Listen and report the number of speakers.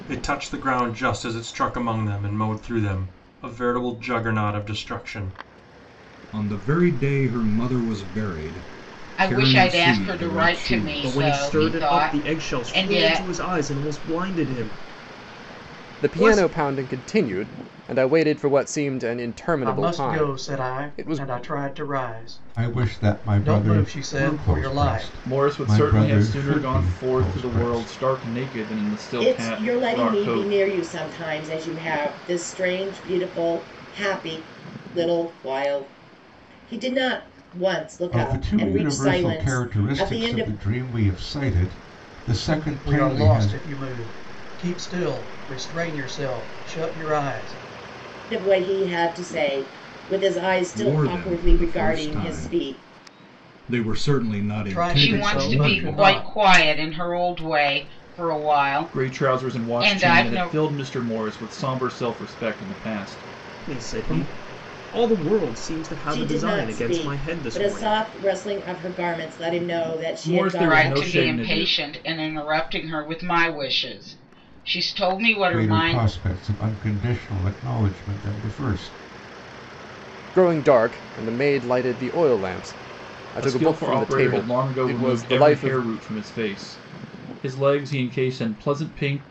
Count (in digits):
9